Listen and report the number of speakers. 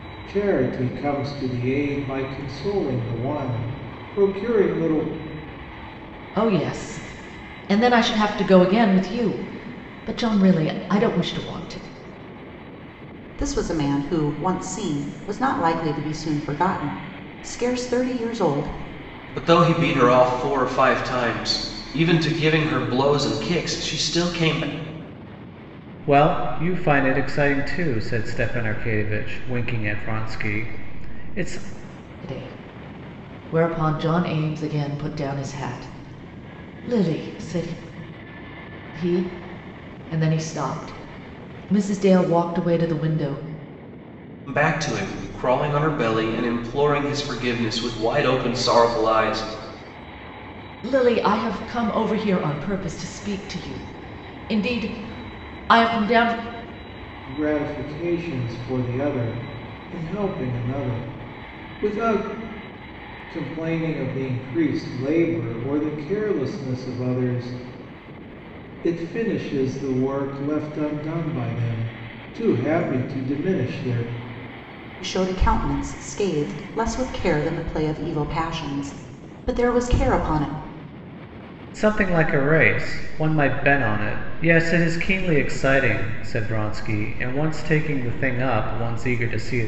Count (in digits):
5